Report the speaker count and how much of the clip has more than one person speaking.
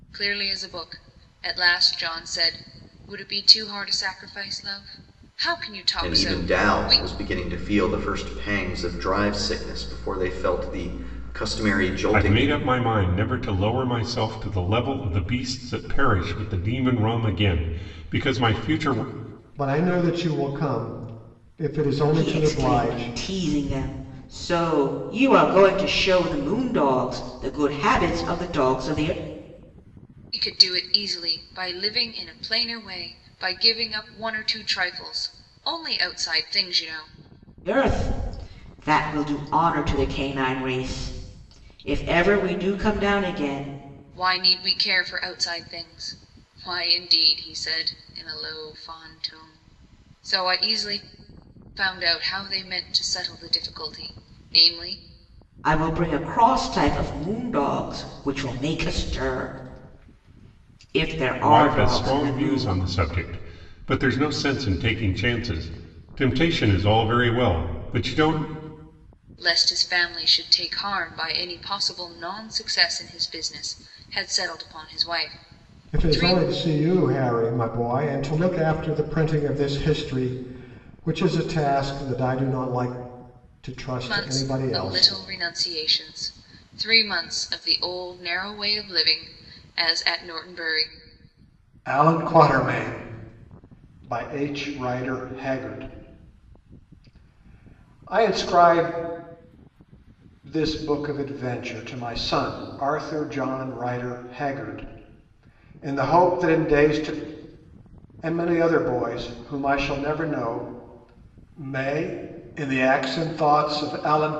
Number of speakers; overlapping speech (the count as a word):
five, about 5%